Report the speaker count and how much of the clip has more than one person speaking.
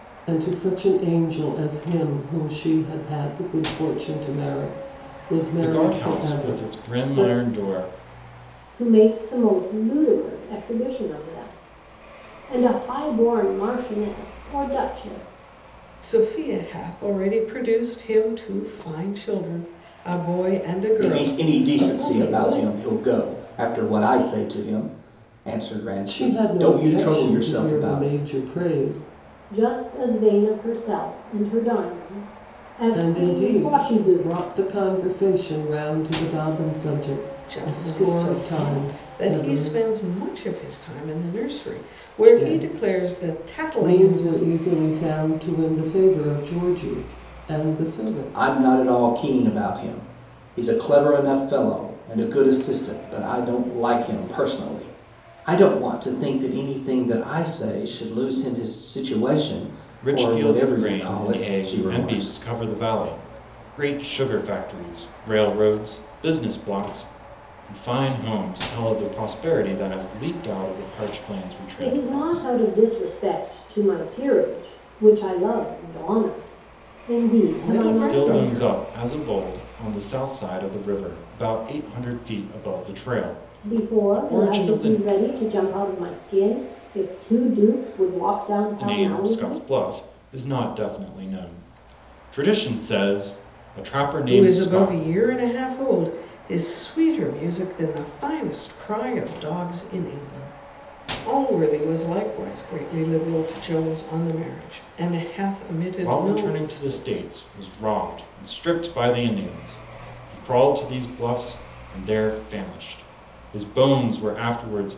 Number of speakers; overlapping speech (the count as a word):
five, about 18%